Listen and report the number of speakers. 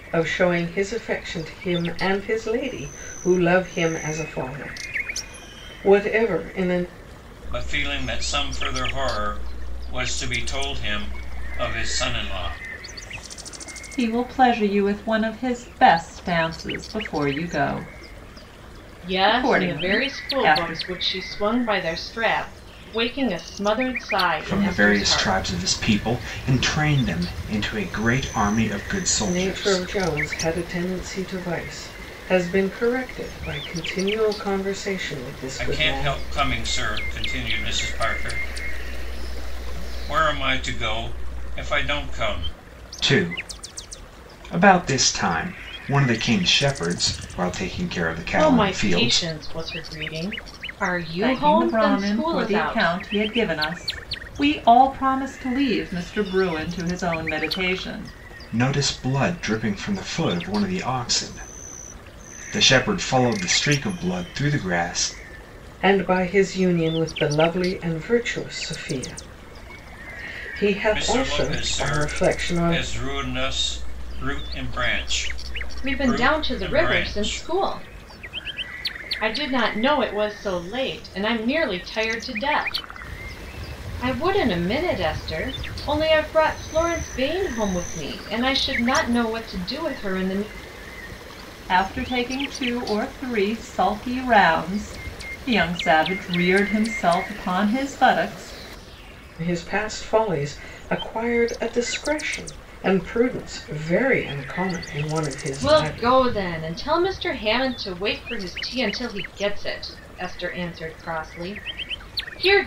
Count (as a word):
five